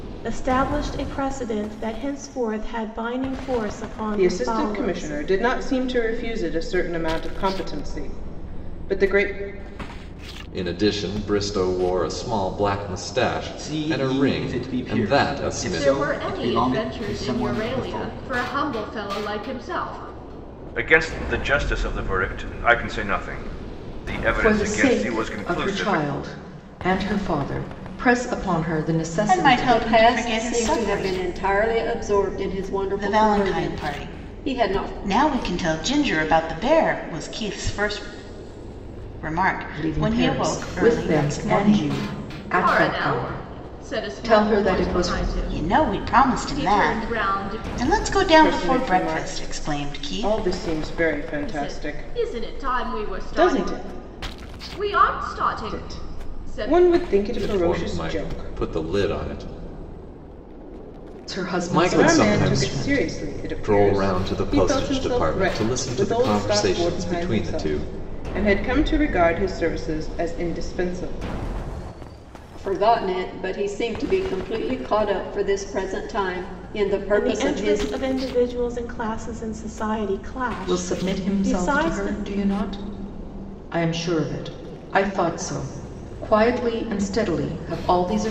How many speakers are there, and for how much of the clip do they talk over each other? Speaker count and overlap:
9, about 38%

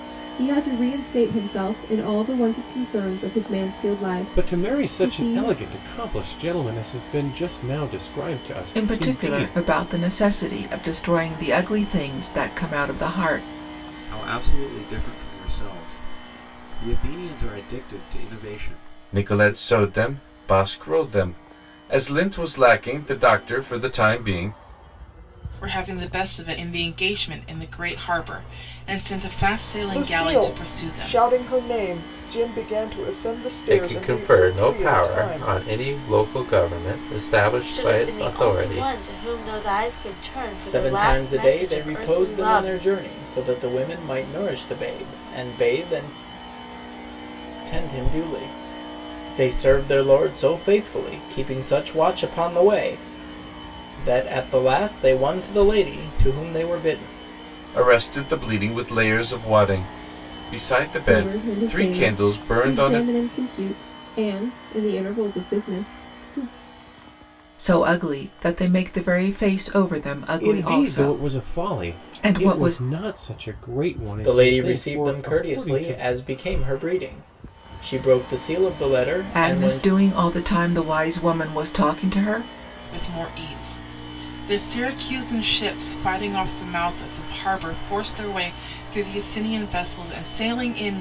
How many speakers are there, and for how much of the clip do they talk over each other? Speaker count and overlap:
10, about 18%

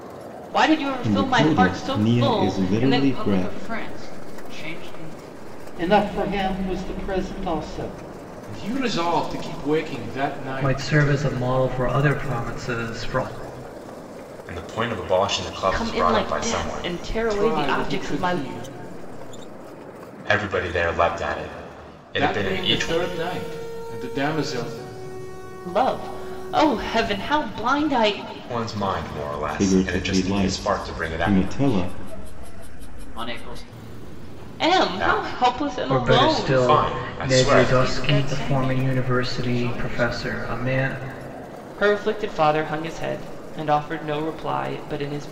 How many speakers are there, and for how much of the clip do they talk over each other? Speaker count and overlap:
7, about 31%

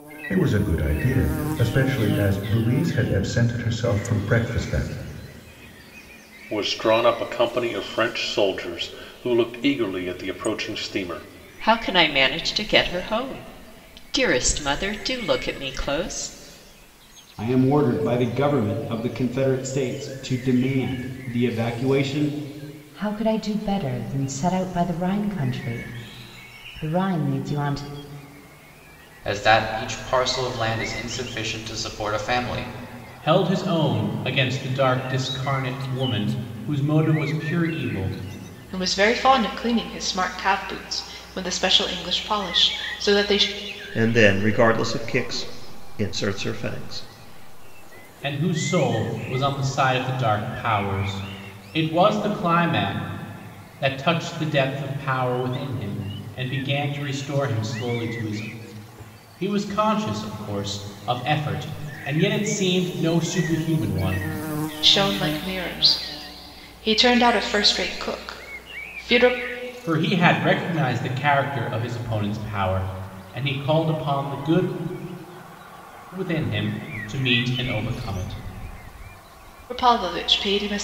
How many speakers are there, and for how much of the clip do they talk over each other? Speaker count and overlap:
9, no overlap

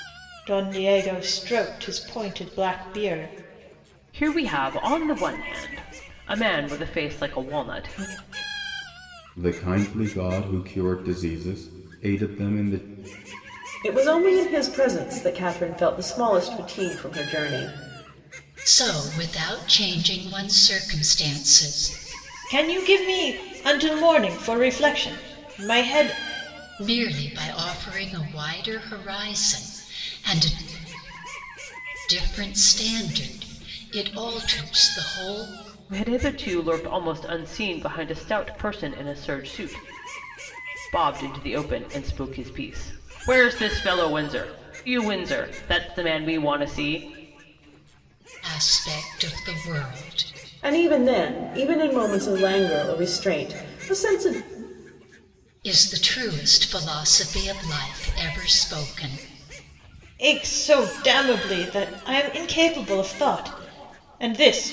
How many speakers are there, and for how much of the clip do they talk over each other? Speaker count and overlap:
5, no overlap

